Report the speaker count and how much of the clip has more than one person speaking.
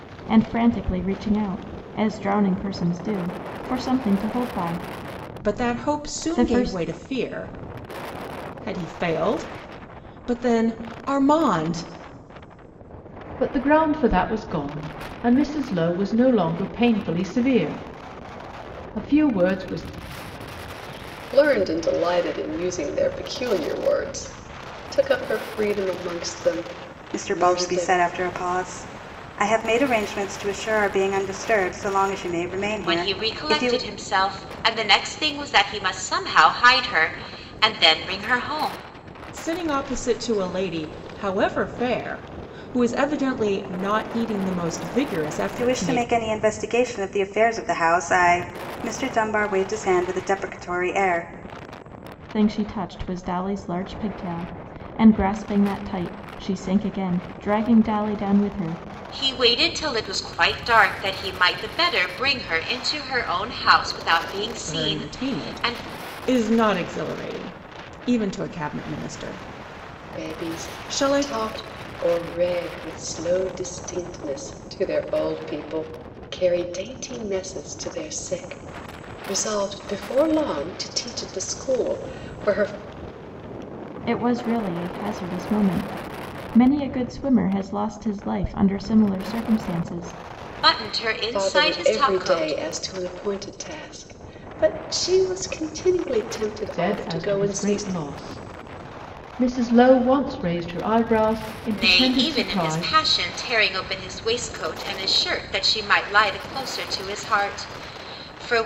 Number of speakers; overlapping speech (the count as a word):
six, about 10%